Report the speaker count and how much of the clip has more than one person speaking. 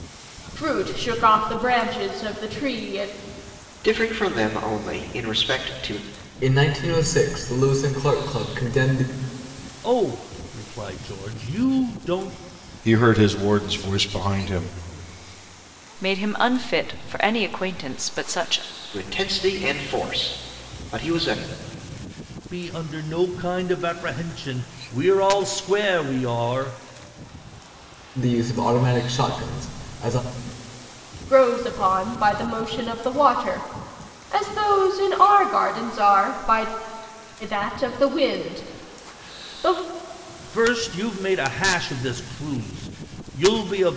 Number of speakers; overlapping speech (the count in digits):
6, no overlap